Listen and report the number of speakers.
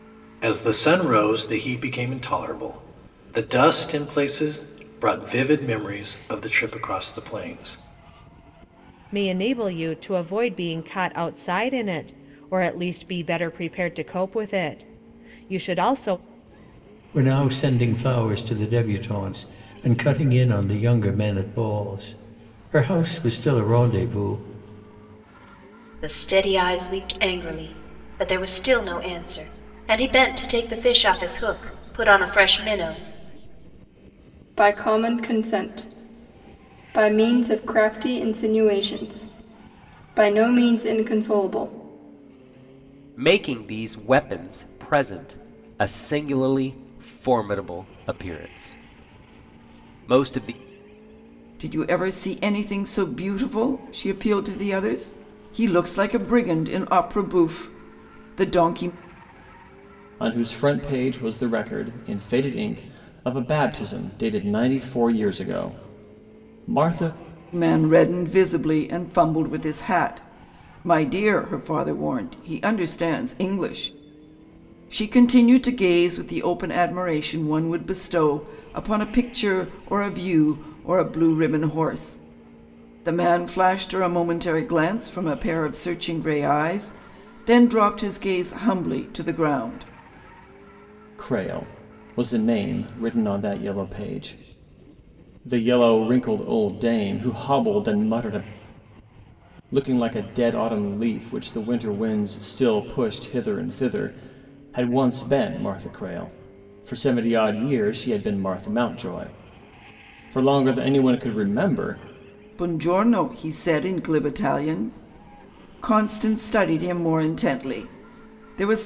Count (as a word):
eight